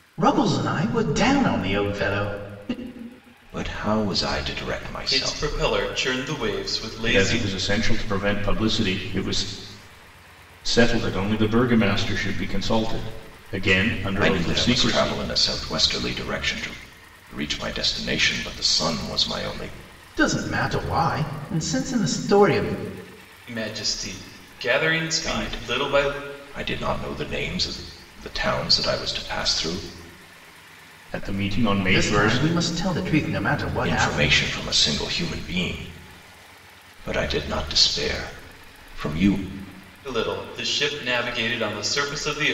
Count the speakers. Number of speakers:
four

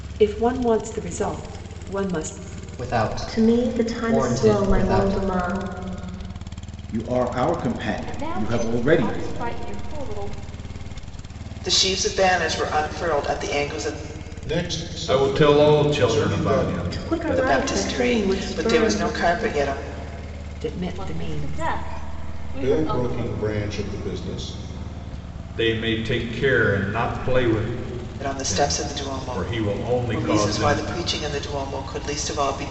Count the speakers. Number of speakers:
eight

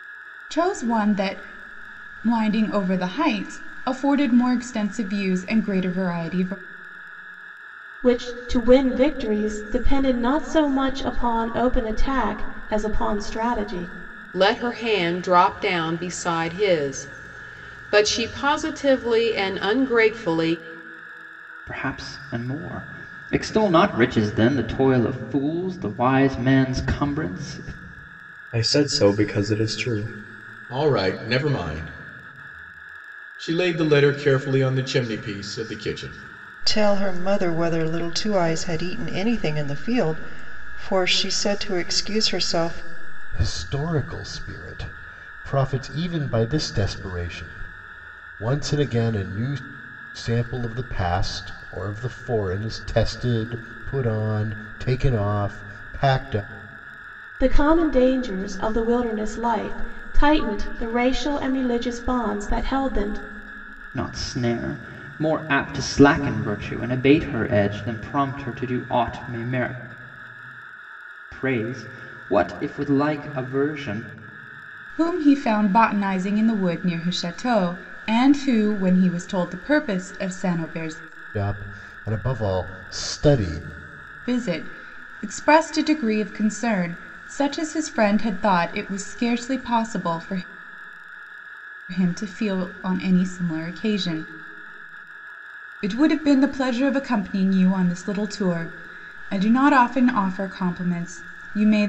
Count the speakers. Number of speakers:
eight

